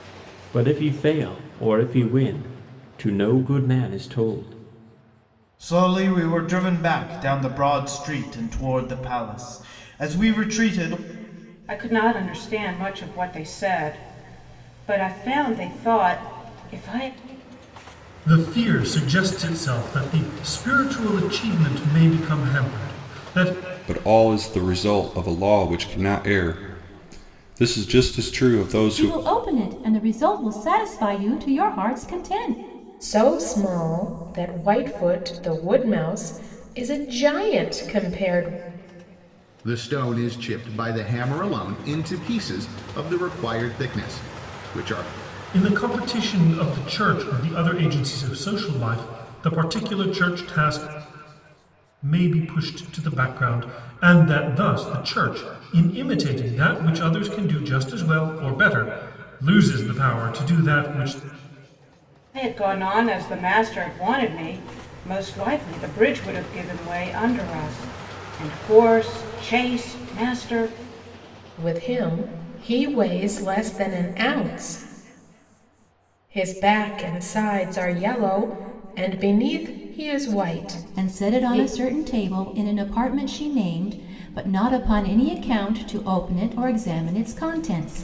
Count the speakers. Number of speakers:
8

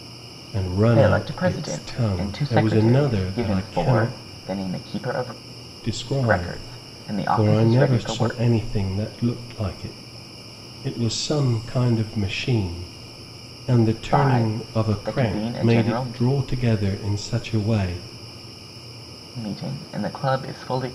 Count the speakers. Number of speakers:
2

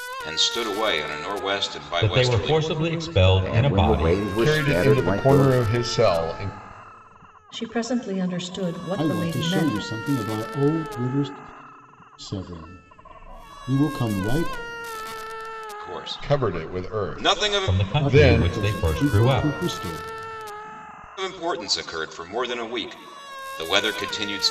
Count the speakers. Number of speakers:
6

